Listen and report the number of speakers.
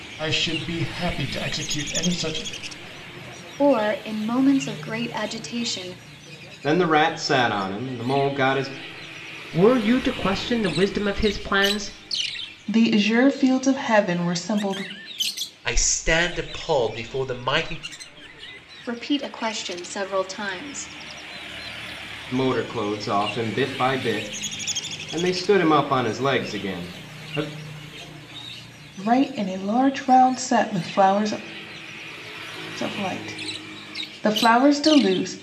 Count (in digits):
6